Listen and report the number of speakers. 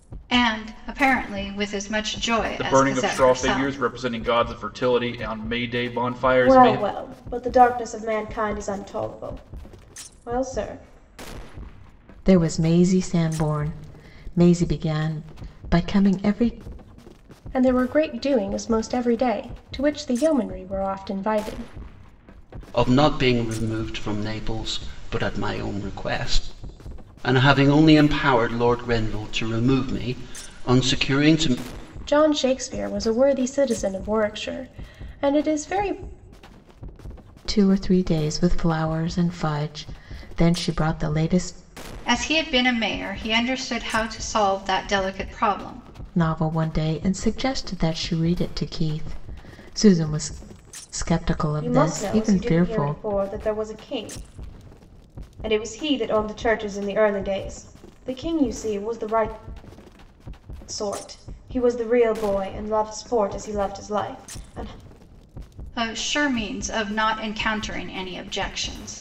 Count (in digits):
6